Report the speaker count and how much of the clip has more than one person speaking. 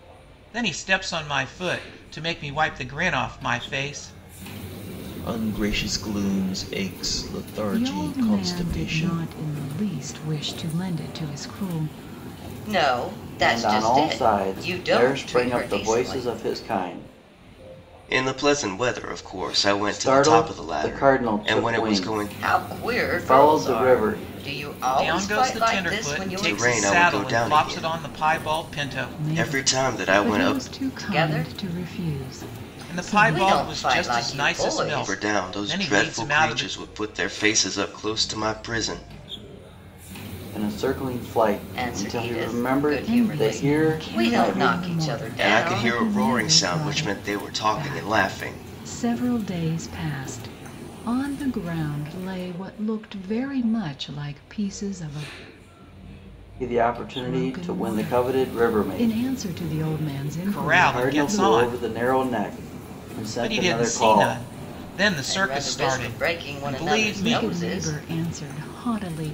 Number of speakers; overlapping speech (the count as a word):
six, about 49%